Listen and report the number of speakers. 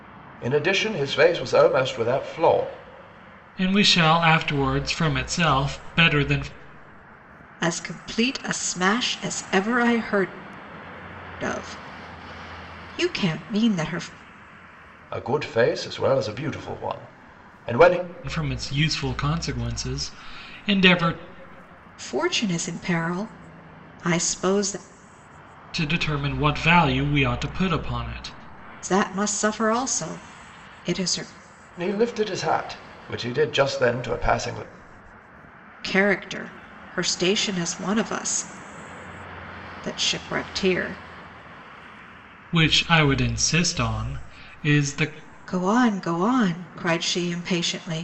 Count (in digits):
3